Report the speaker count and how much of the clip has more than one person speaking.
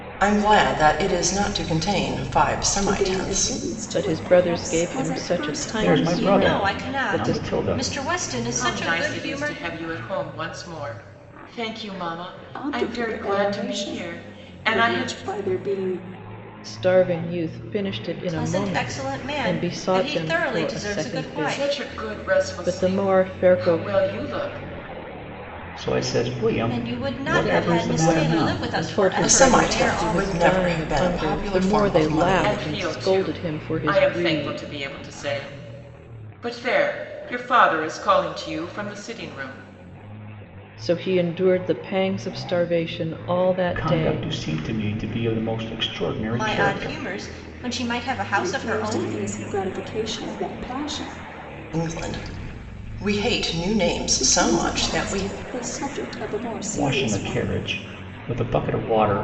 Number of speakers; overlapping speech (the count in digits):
6, about 44%